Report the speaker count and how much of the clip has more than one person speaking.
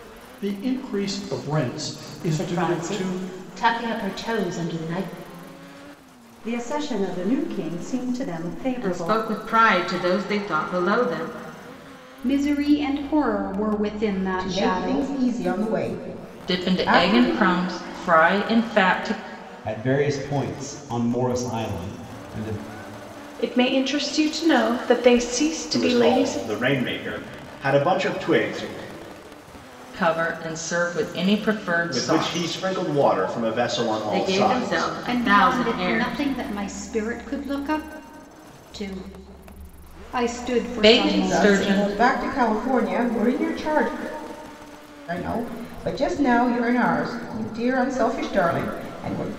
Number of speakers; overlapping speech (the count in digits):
10, about 16%